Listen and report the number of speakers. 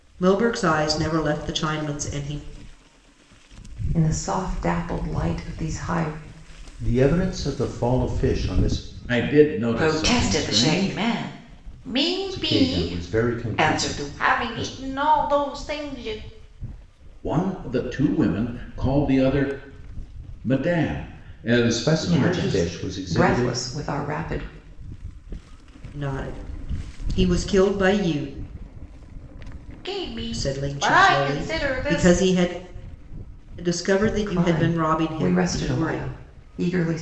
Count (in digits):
5